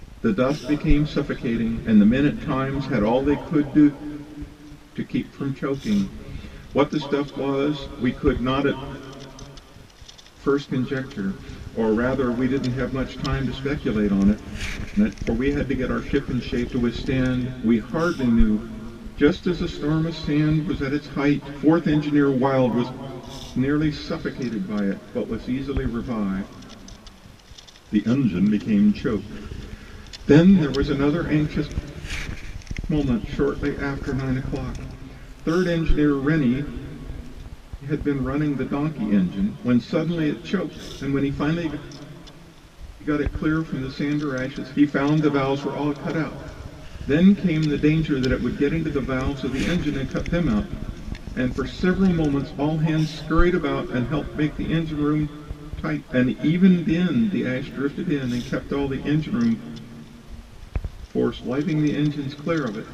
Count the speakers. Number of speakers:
1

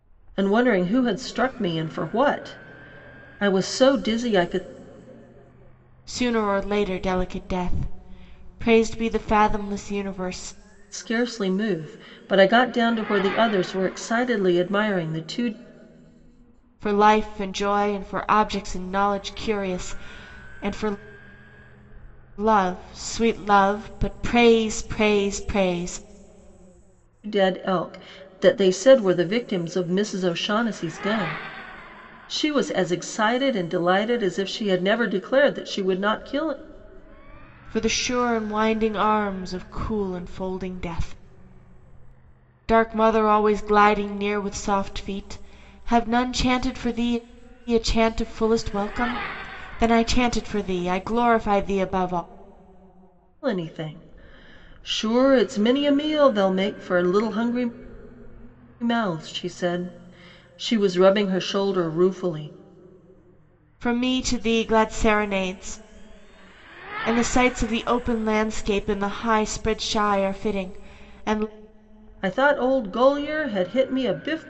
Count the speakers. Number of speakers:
2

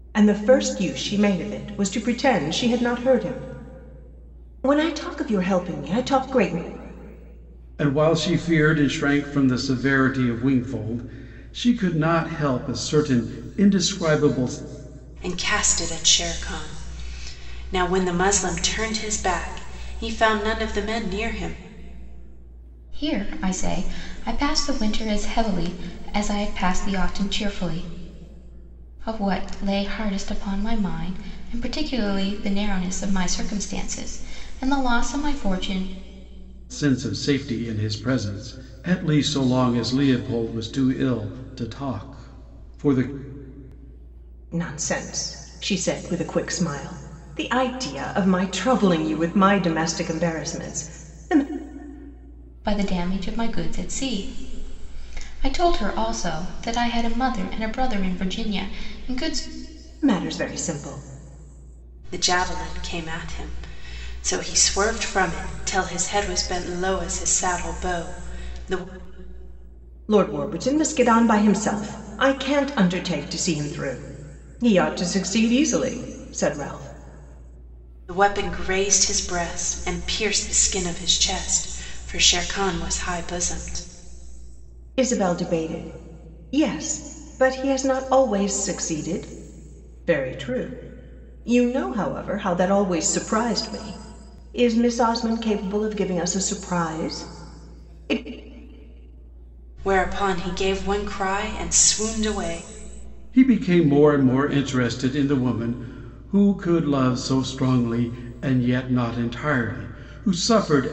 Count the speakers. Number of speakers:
4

